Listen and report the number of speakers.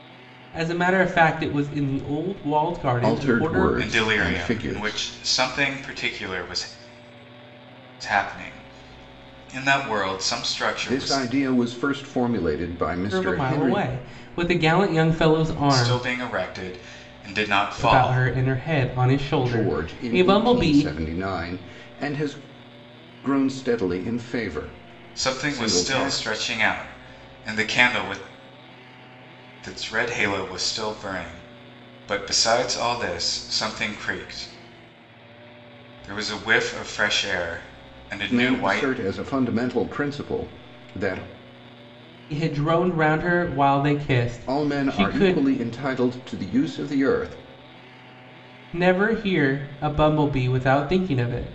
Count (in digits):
3